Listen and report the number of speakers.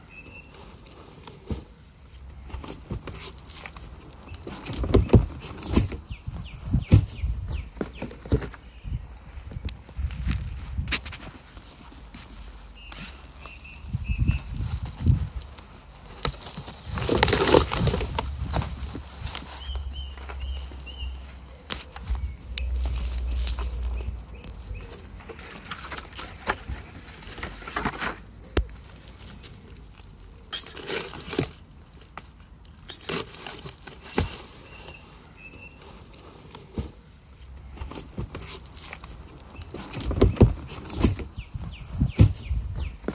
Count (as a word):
zero